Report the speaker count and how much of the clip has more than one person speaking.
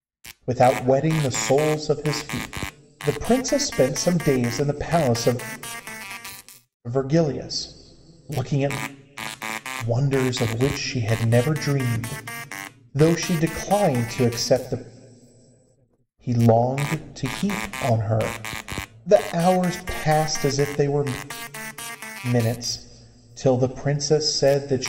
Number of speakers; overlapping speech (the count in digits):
1, no overlap